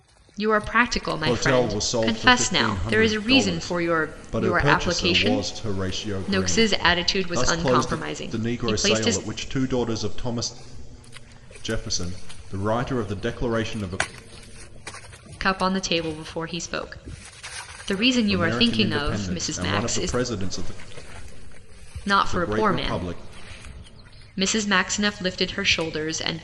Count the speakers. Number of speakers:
2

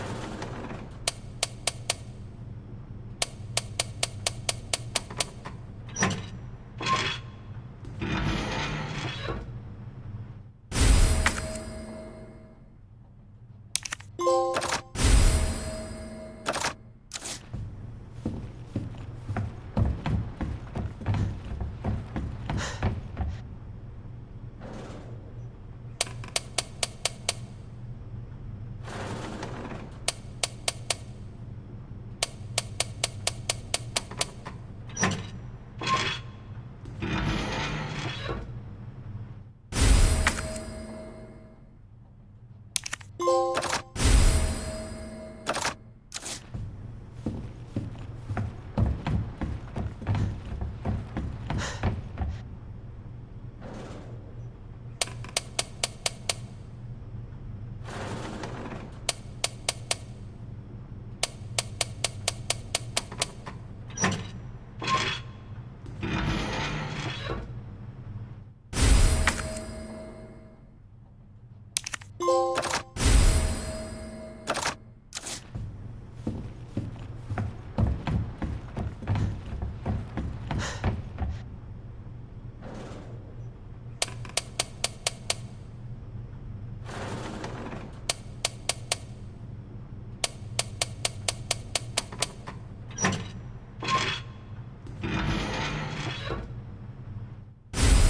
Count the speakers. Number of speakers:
0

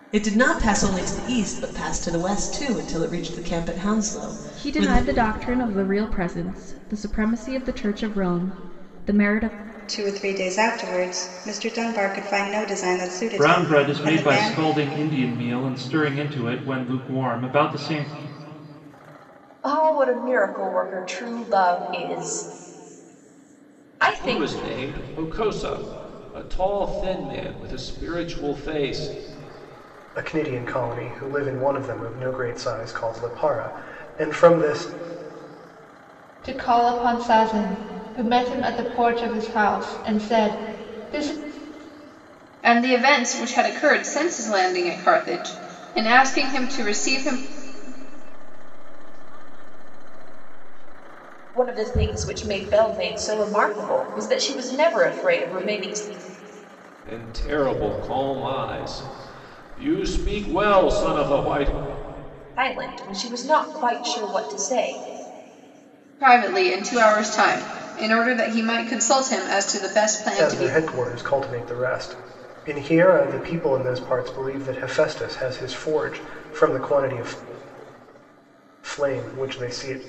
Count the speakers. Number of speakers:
10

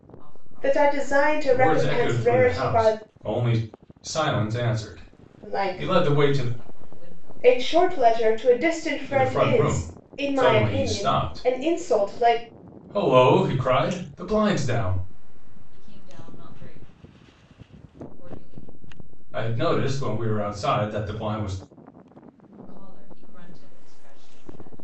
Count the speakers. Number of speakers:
3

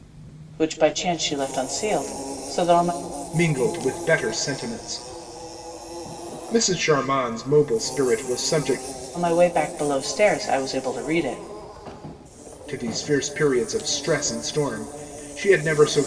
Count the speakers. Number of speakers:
2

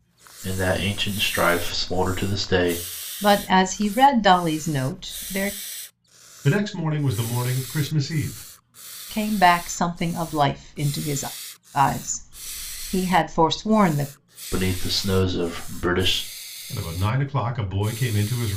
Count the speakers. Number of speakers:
3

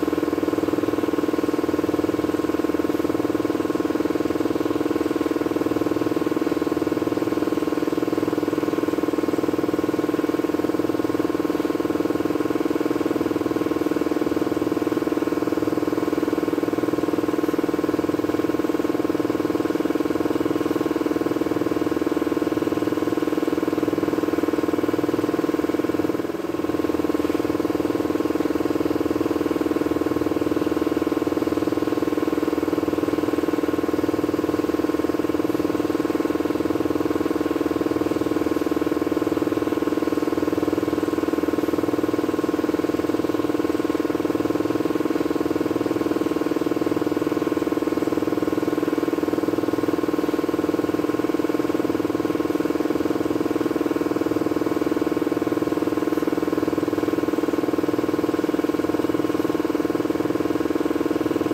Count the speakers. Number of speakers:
0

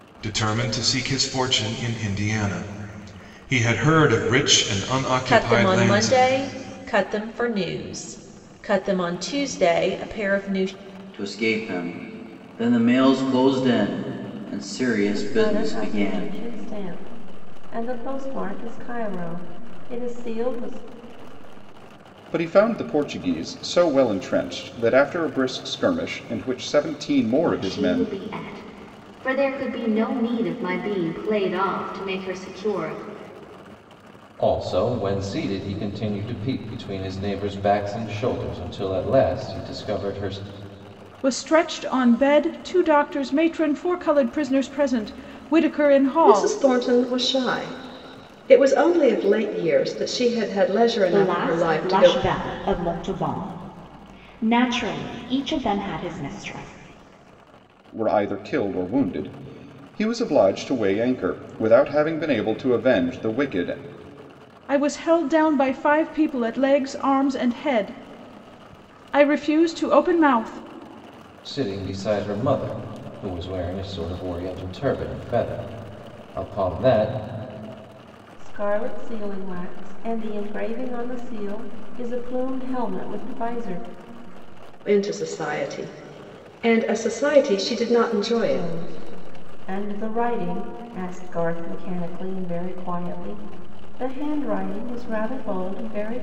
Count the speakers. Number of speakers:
10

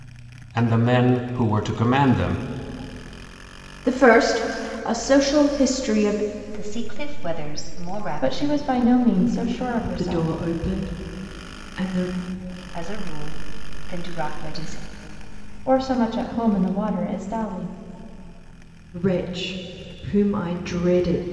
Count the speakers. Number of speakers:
5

